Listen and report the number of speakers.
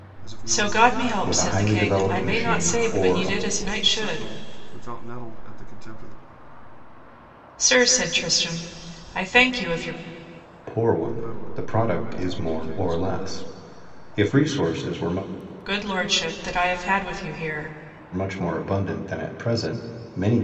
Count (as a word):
three